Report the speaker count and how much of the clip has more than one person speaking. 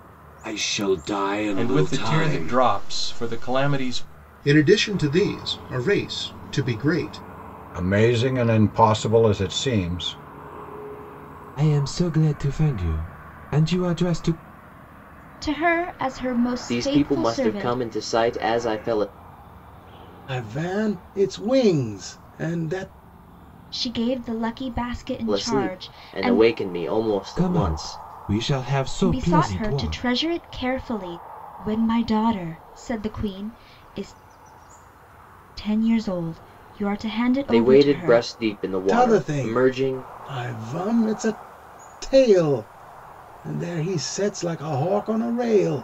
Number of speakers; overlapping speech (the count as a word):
eight, about 16%